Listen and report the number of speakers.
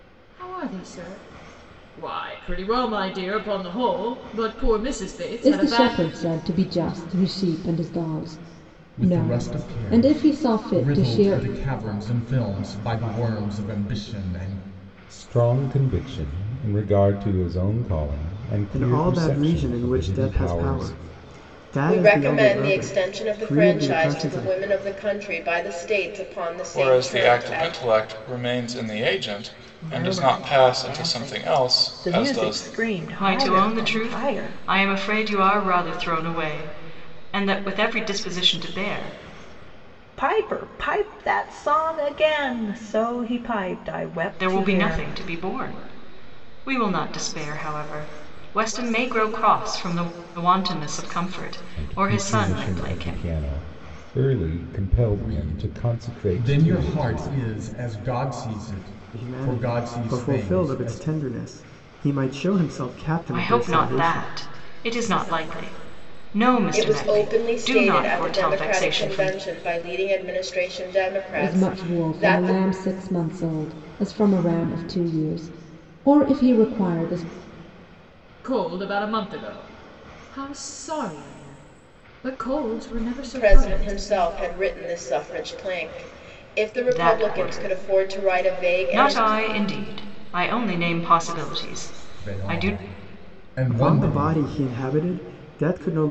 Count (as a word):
nine